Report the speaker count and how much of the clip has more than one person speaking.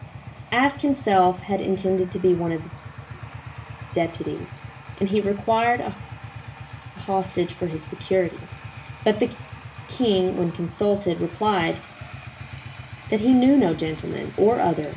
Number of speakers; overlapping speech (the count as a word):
one, no overlap